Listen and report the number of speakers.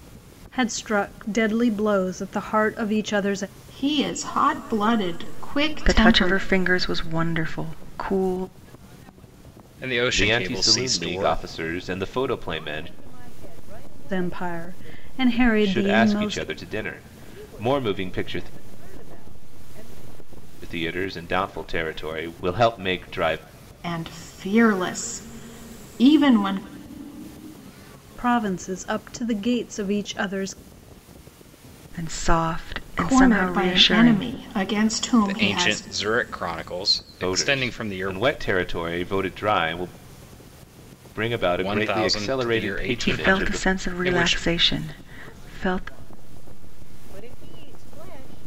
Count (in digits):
6